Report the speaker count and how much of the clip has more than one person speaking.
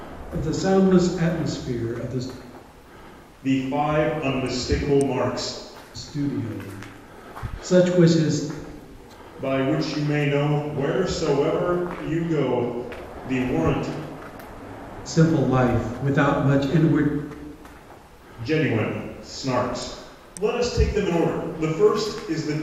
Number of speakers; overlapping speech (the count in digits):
2, no overlap